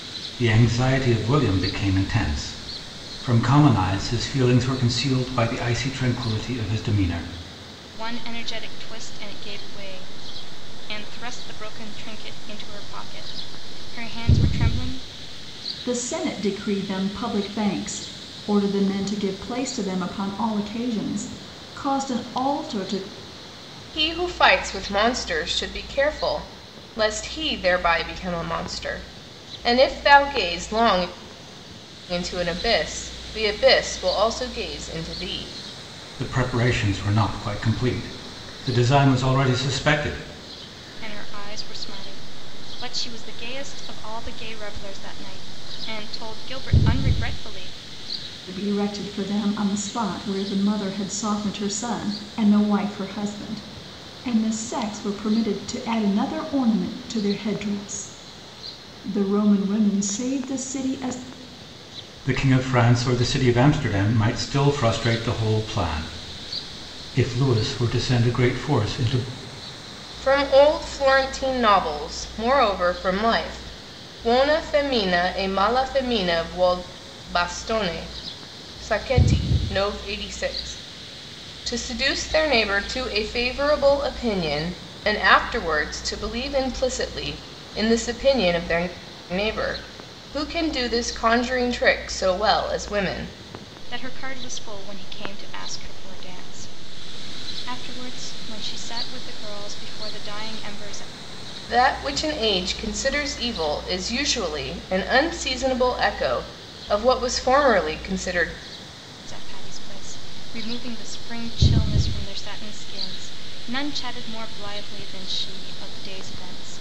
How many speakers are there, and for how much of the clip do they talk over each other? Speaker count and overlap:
4, no overlap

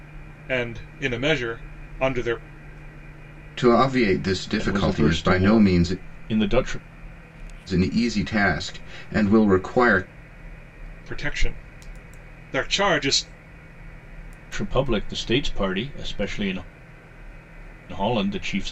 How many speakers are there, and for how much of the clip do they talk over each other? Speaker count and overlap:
3, about 8%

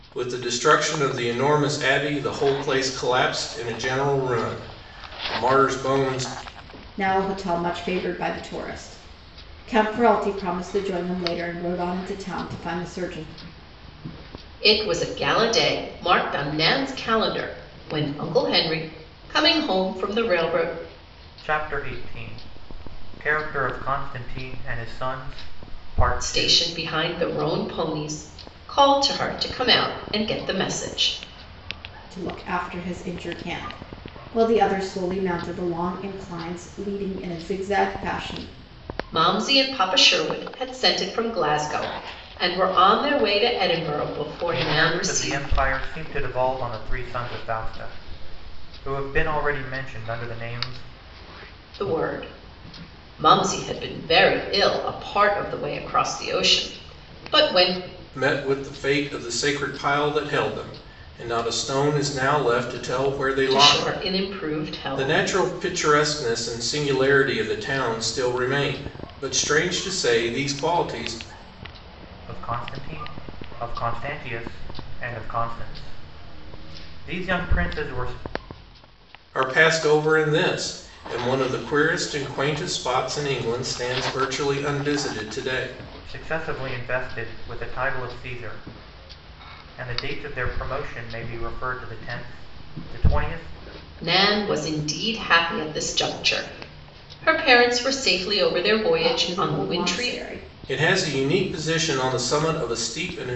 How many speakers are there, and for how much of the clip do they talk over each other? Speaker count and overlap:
4, about 3%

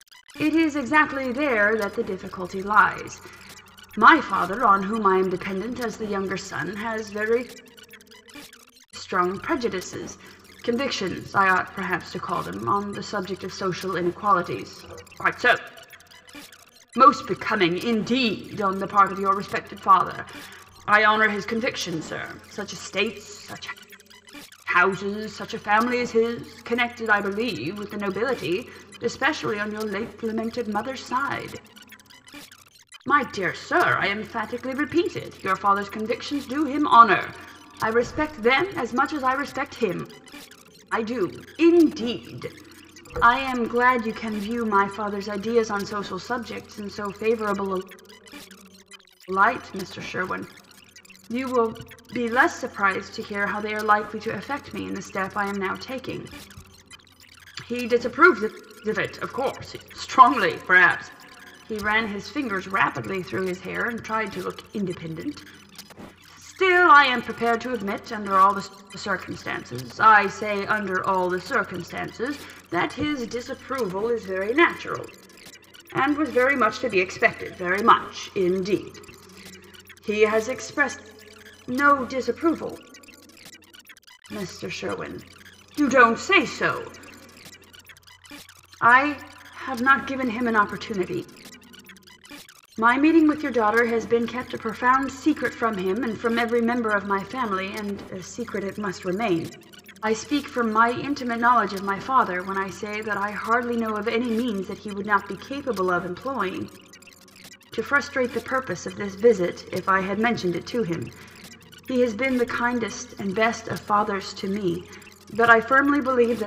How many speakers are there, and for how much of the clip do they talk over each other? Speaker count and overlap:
1, no overlap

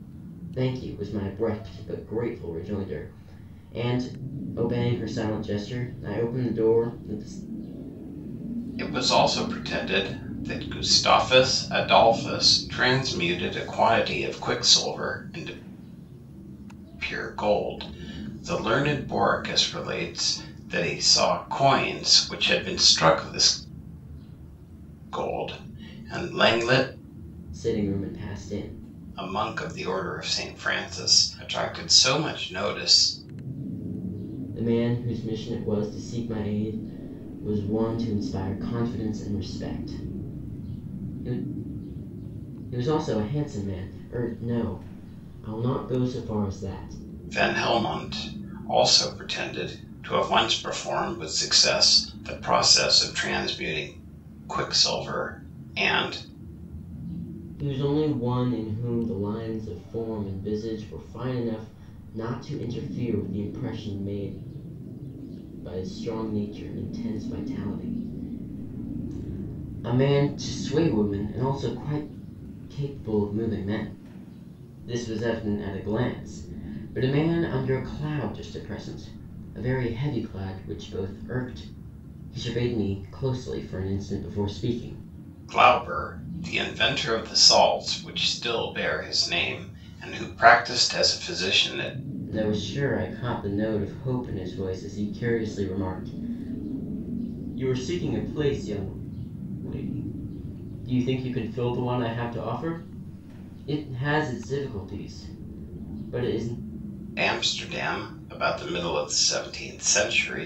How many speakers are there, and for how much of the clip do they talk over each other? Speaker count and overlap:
2, no overlap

